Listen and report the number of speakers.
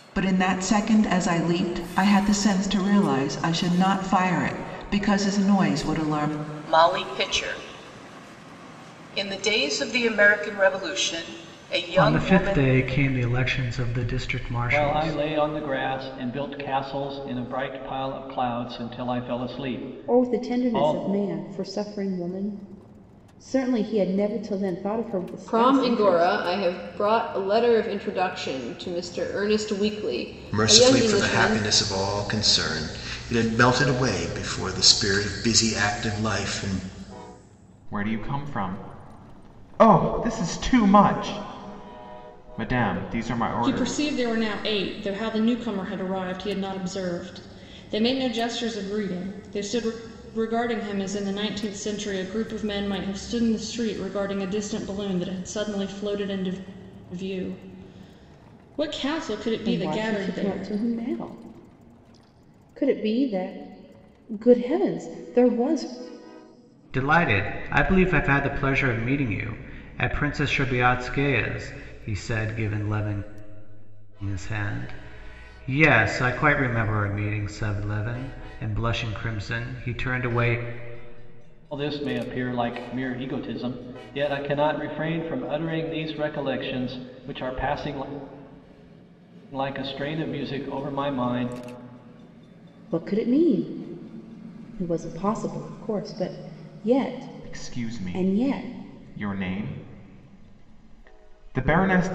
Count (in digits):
9